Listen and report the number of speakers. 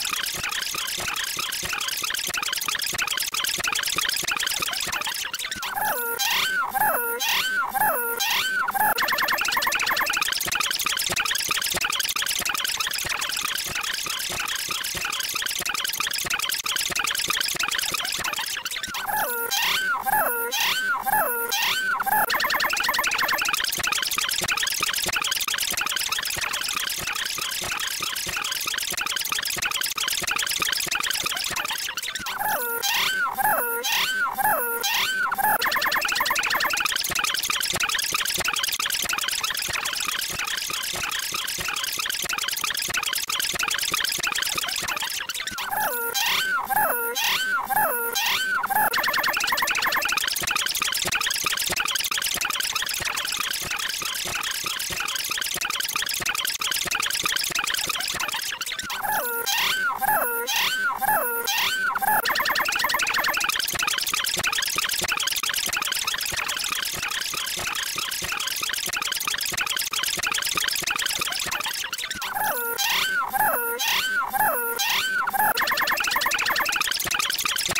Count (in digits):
0